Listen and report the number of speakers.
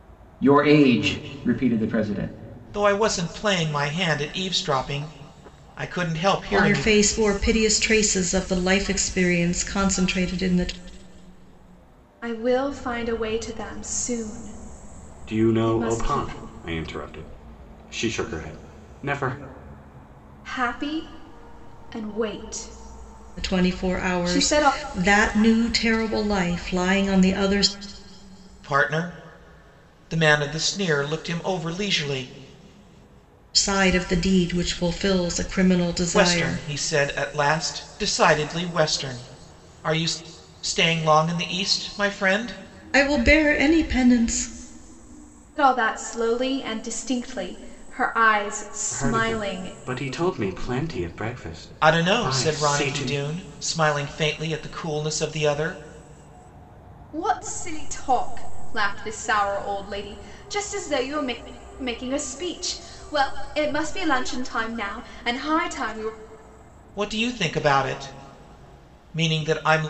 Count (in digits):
5